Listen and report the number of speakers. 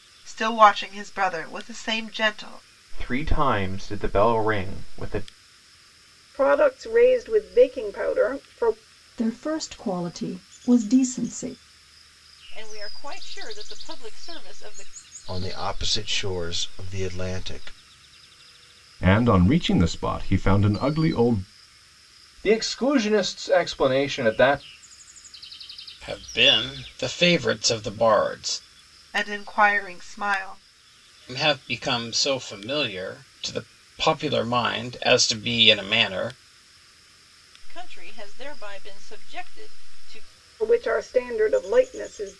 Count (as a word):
nine